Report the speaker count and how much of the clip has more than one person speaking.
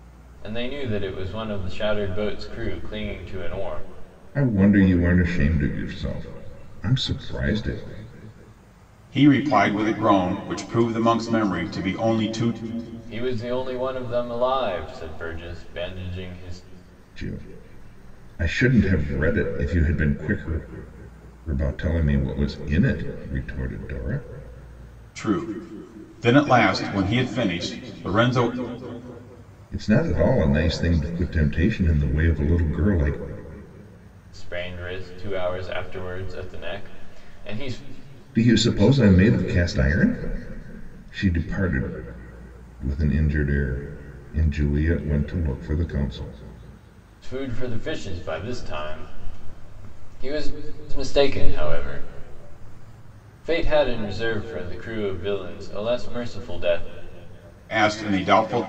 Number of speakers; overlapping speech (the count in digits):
3, no overlap